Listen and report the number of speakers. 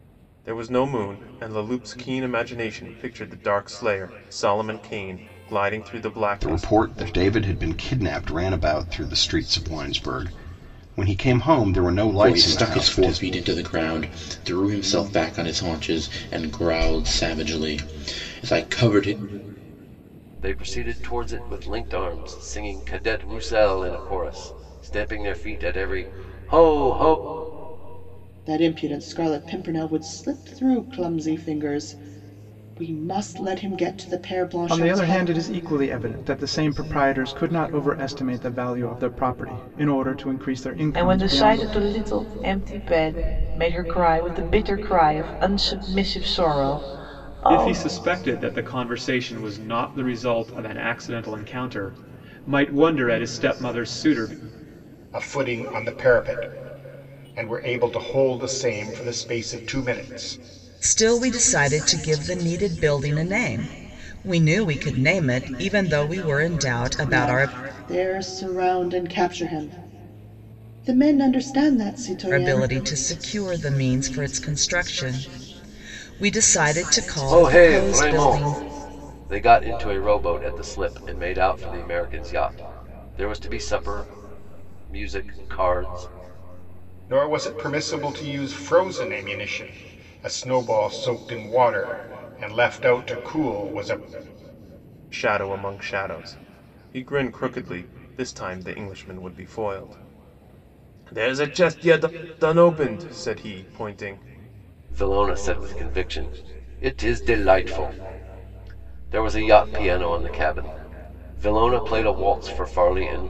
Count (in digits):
10